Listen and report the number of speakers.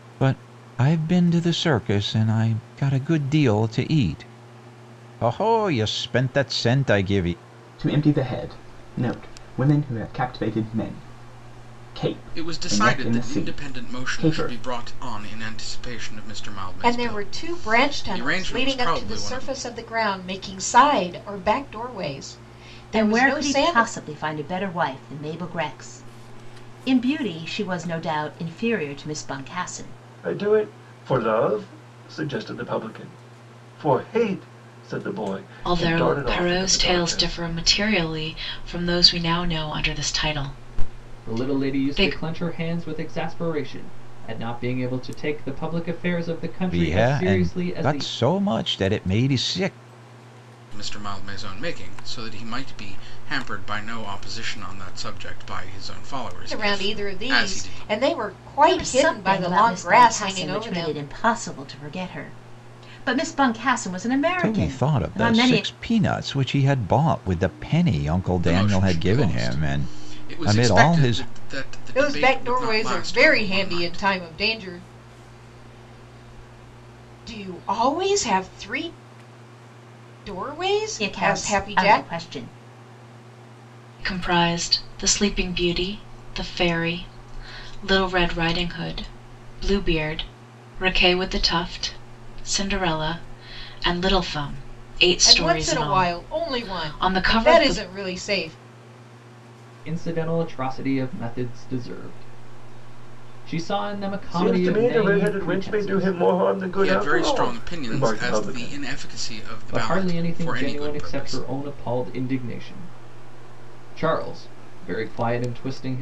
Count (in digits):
8